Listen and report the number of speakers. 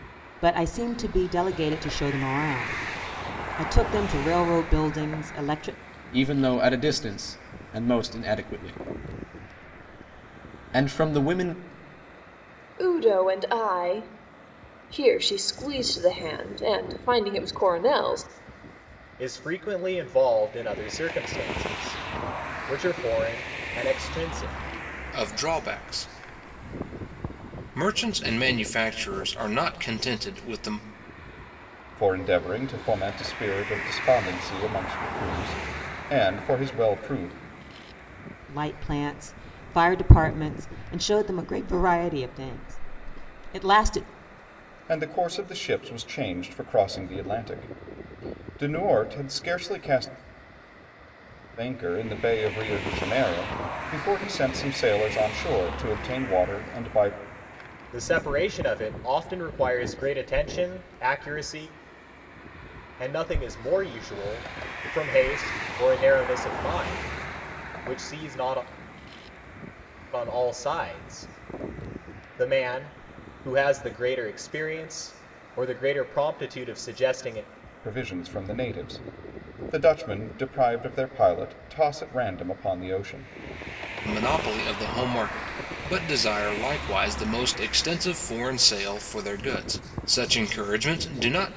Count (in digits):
6